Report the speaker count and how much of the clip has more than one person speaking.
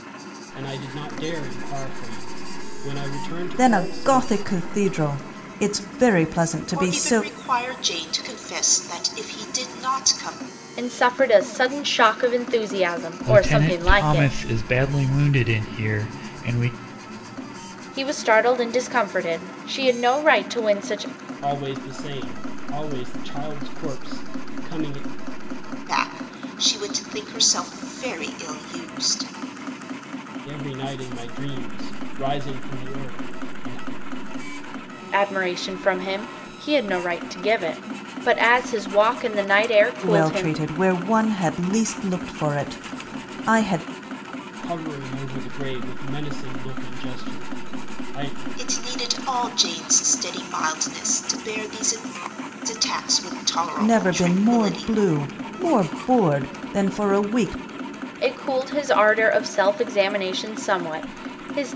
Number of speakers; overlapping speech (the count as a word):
five, about 7%